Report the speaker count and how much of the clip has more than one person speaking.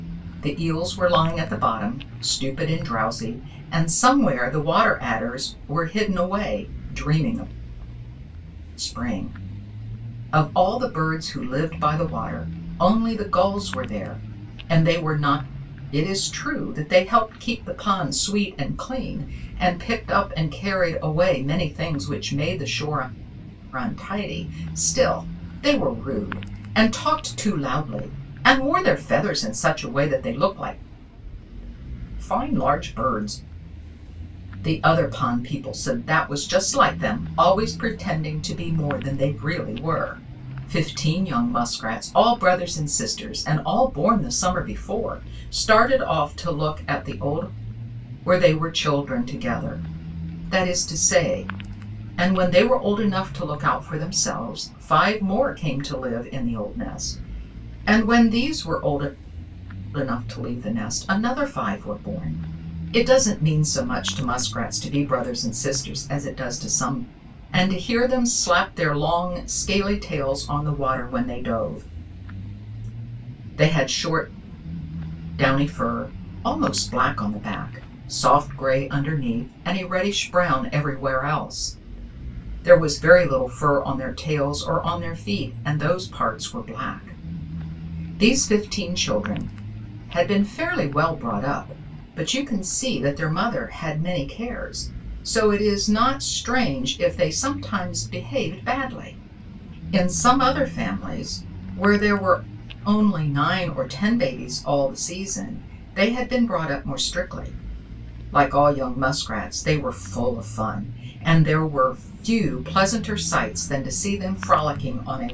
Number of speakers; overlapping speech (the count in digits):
1, no overlap